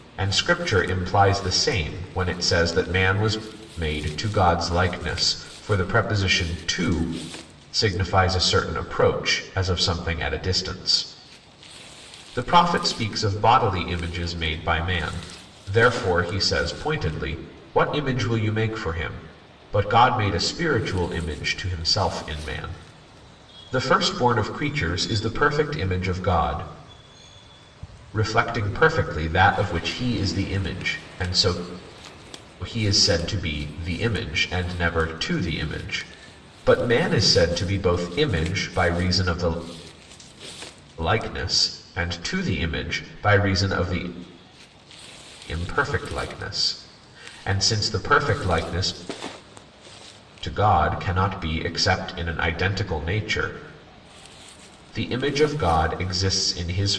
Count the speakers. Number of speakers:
1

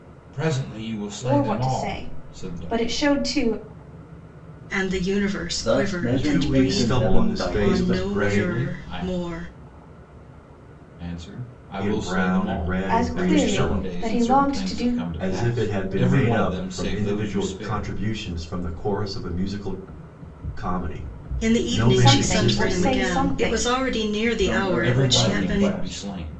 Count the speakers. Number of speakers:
5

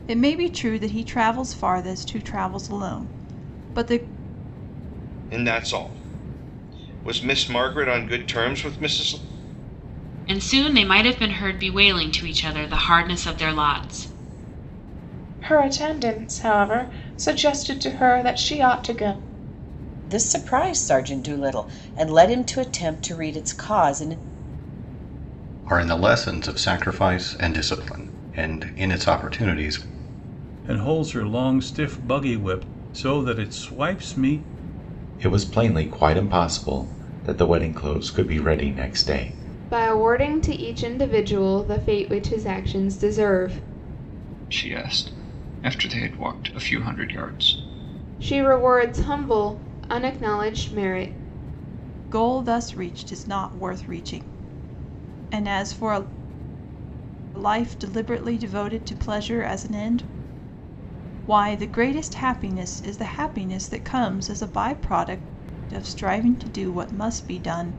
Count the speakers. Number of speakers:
10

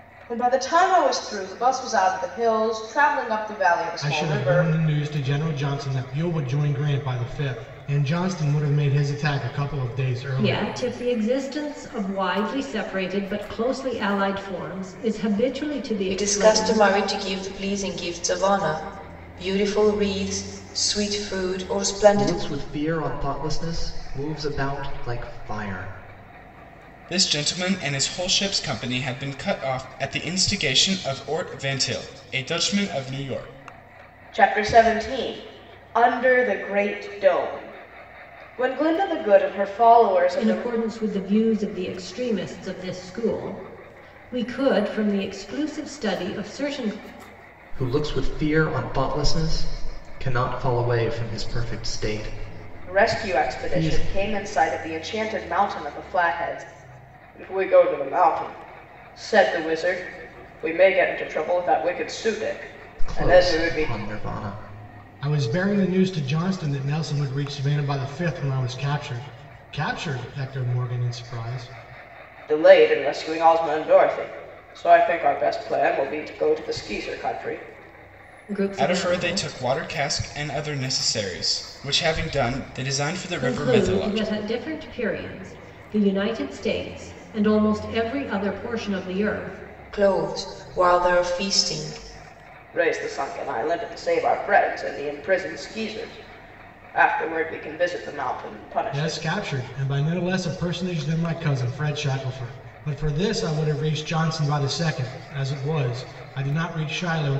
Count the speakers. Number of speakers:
6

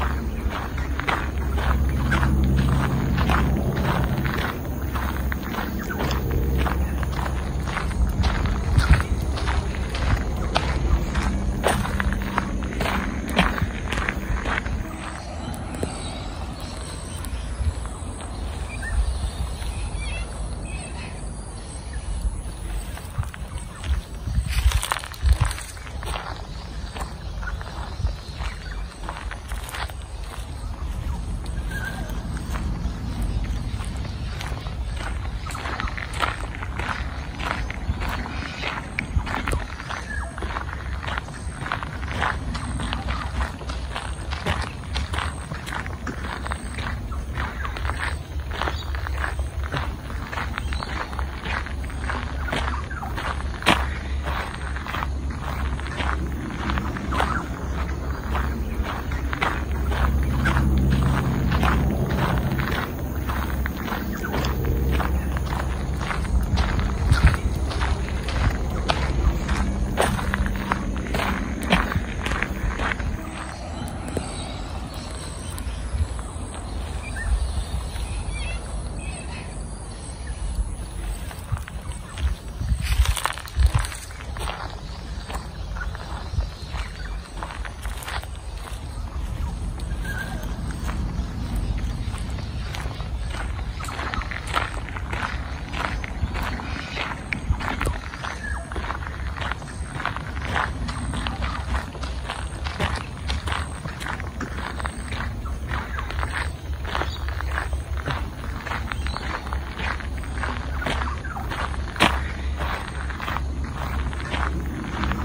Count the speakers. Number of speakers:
0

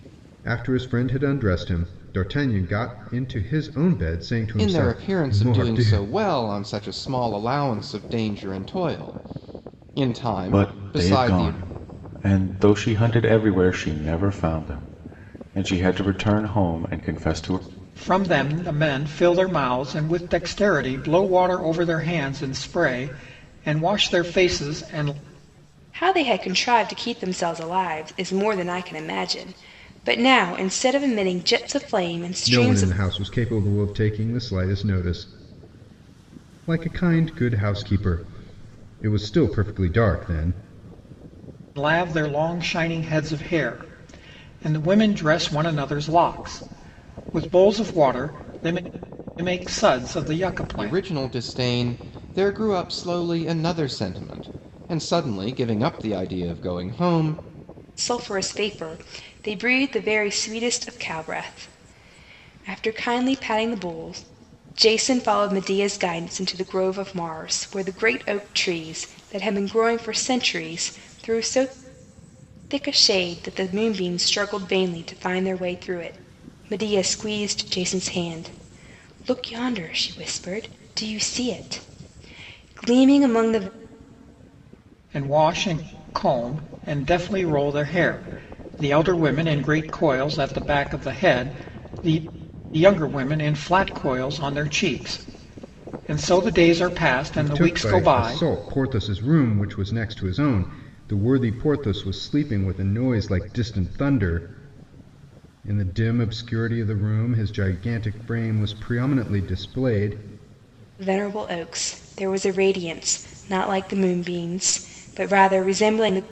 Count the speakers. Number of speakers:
5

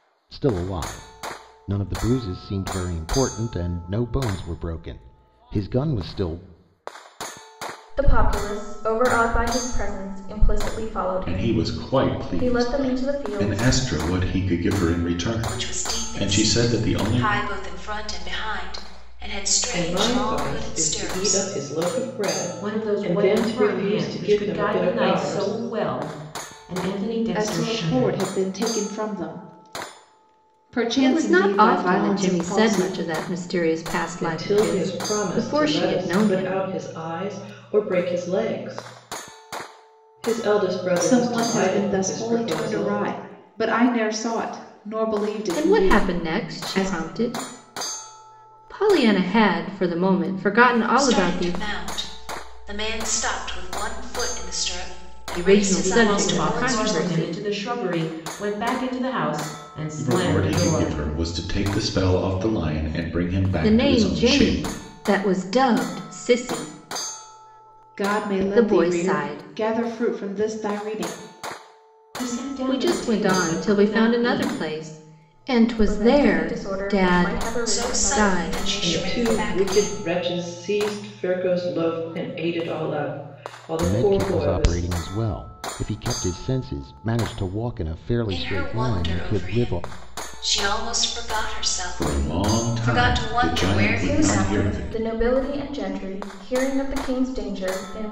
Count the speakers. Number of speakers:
8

